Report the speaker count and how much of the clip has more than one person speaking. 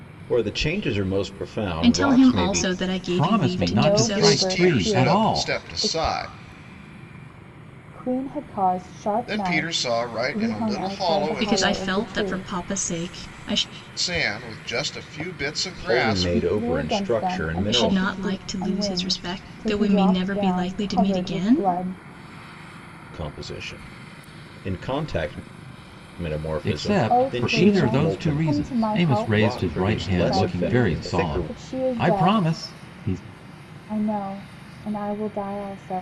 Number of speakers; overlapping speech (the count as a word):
five, about 52%